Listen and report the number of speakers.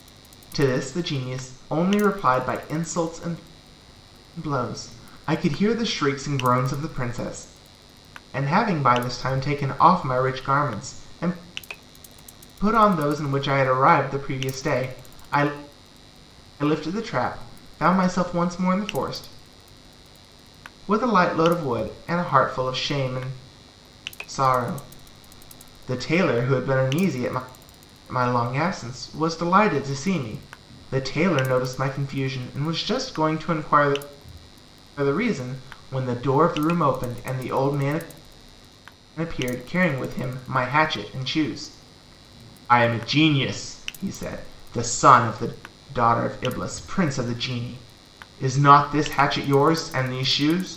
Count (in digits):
1